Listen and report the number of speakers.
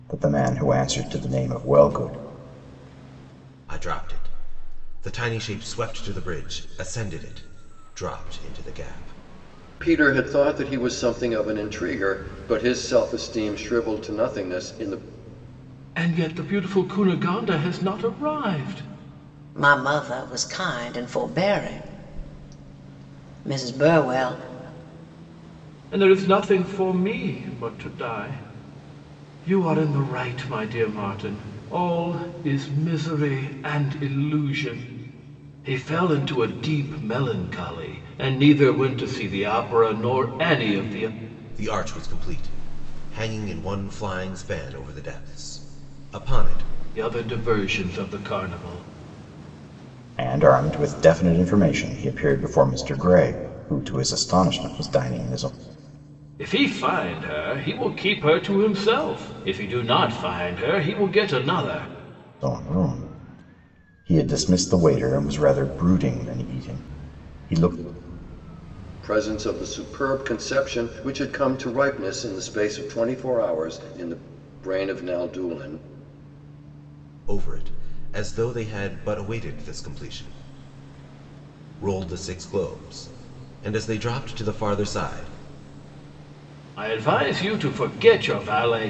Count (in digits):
5